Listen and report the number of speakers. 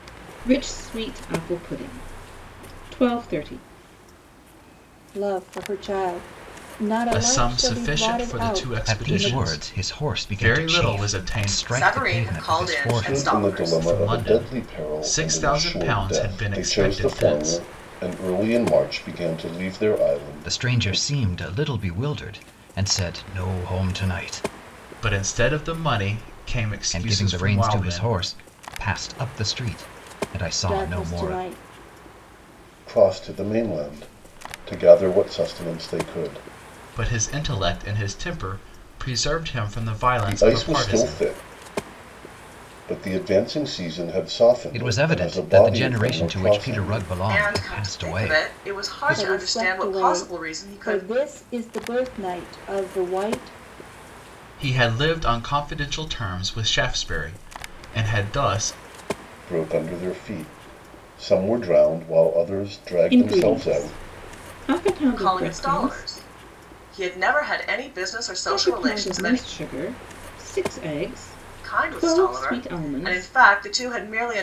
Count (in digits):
6